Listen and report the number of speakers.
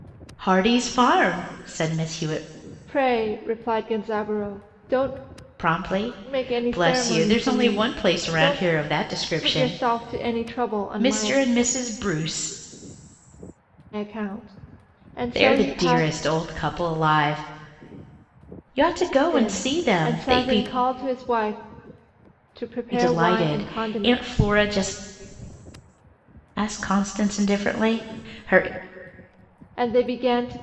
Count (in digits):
2